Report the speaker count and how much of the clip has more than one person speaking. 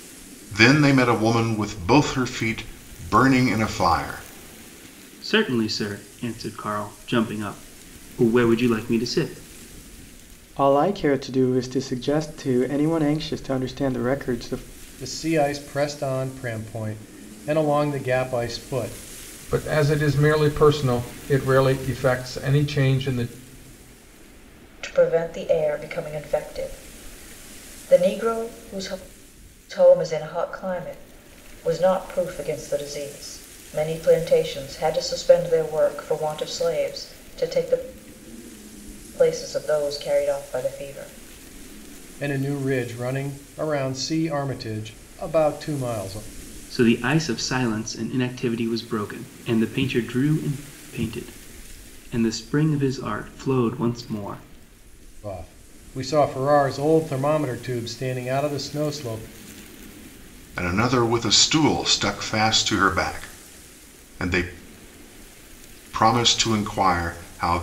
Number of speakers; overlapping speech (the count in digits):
6, no overlap